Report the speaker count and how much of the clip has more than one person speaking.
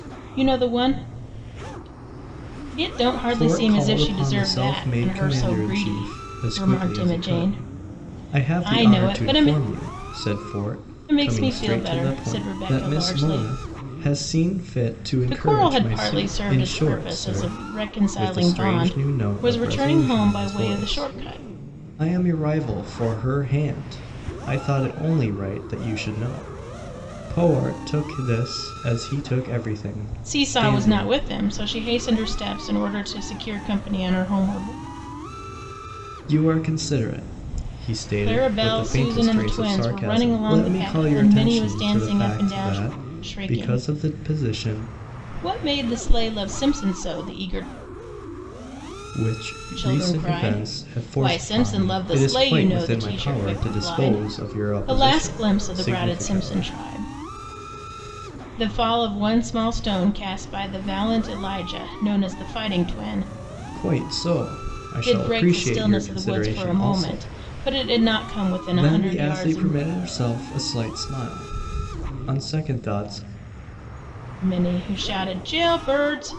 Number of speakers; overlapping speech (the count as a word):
two, about 40%